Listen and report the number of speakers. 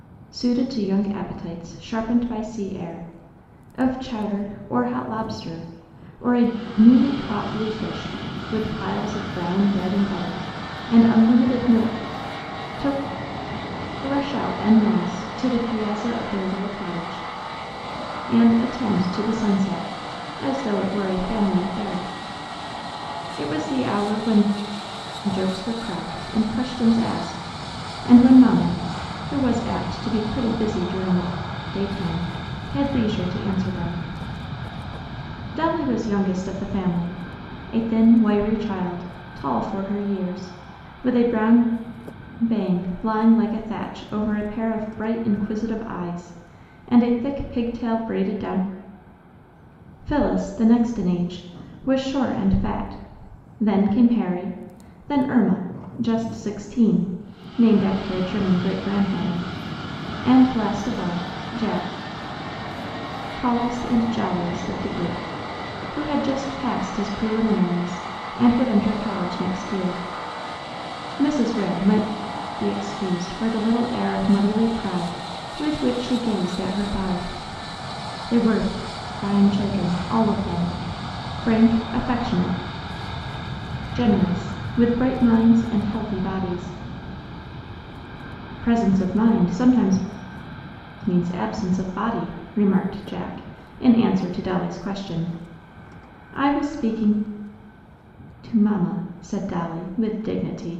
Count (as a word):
one